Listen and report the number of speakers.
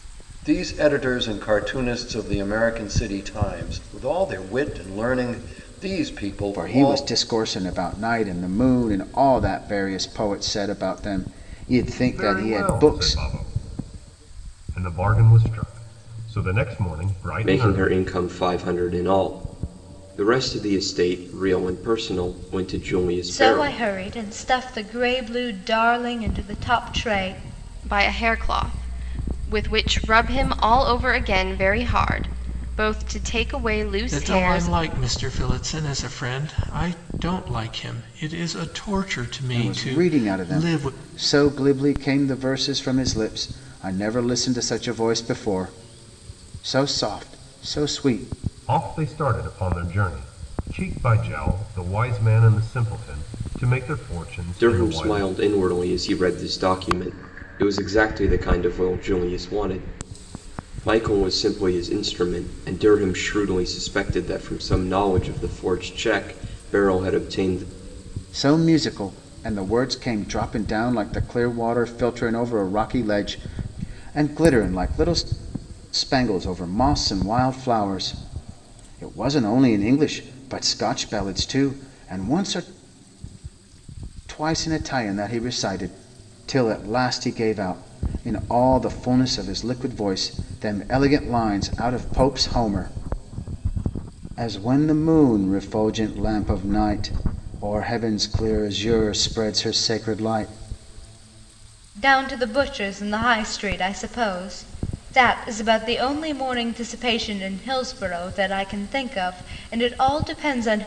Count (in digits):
7